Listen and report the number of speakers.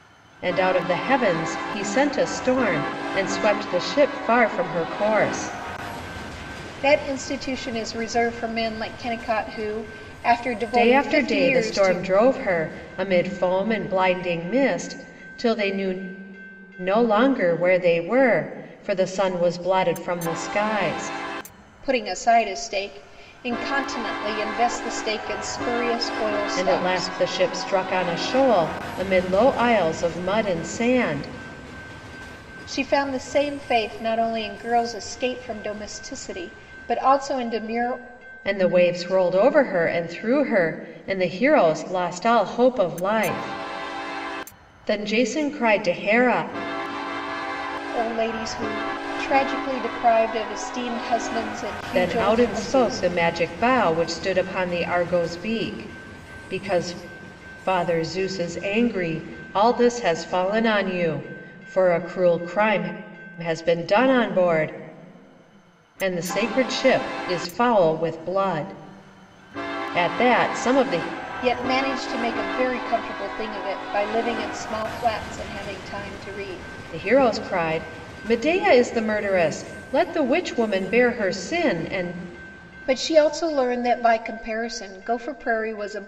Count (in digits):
2